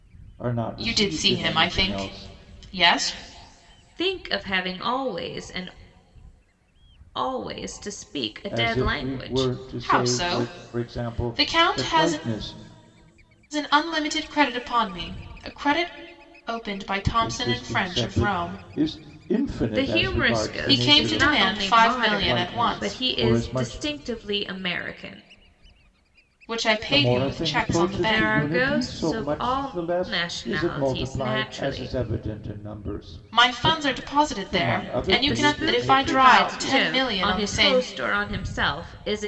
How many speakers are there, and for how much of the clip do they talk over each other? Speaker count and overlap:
three, about 49%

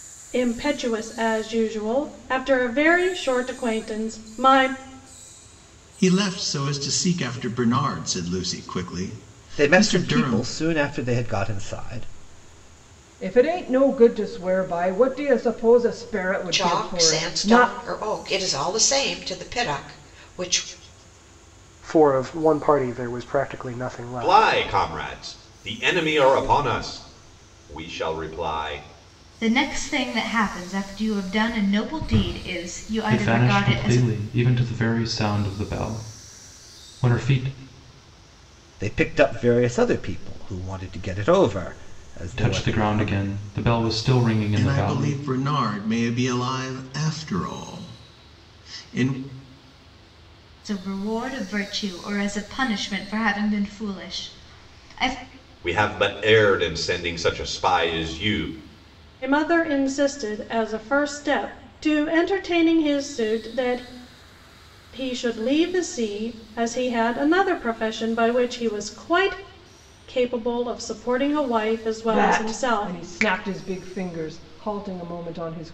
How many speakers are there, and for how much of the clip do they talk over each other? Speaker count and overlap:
nine, about 8%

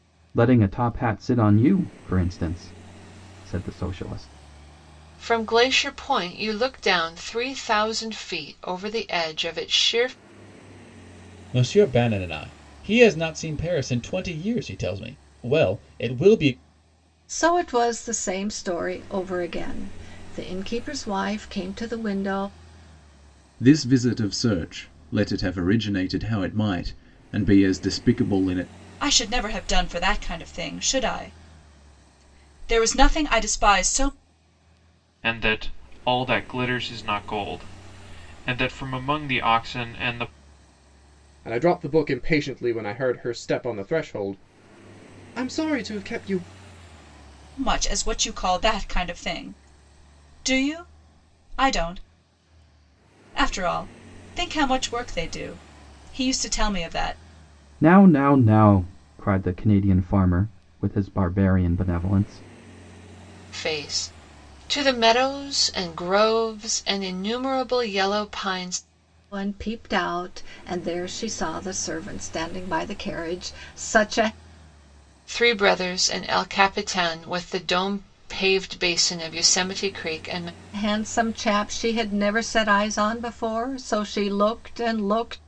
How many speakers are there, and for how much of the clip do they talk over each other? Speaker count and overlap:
eight, no overlap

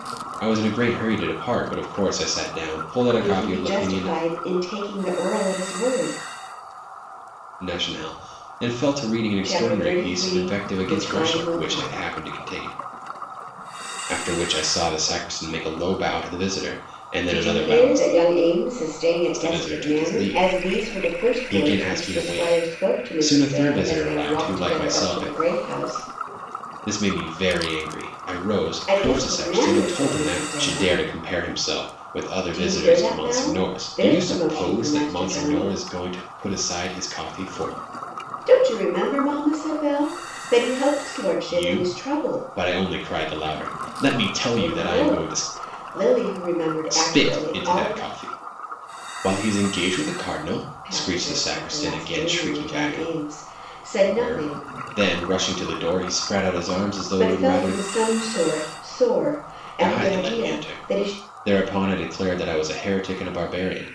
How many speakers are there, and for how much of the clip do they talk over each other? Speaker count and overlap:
two, about 36%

